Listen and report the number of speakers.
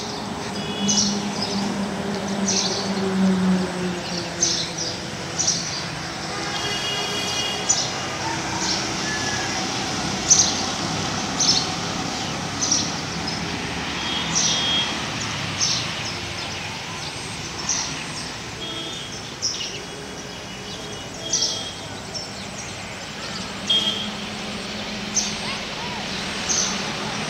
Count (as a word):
zero